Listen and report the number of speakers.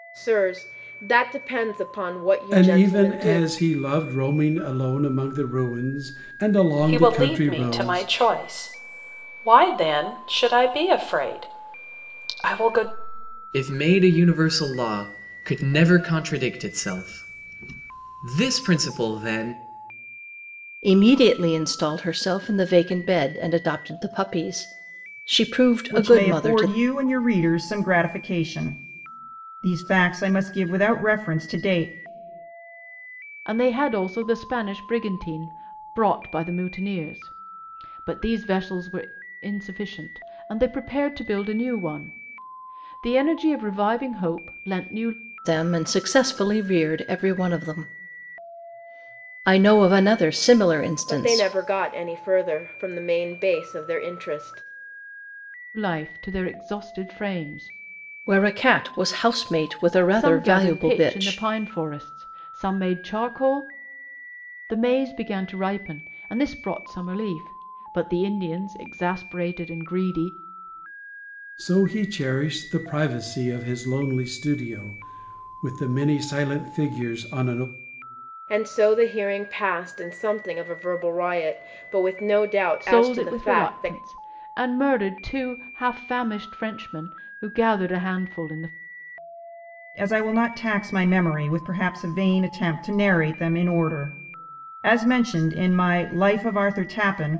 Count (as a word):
seven